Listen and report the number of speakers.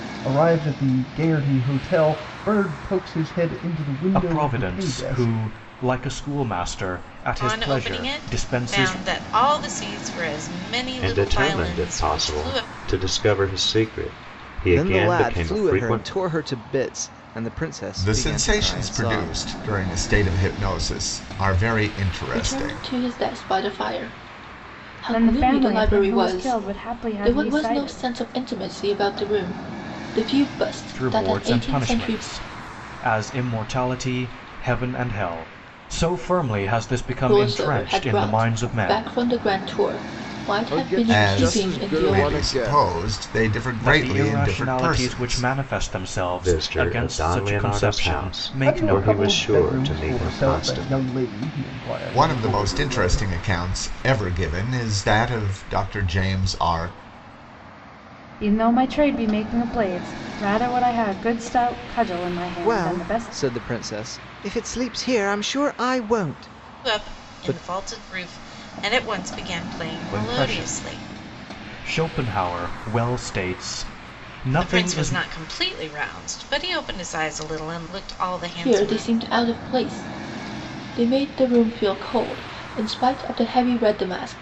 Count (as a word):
eight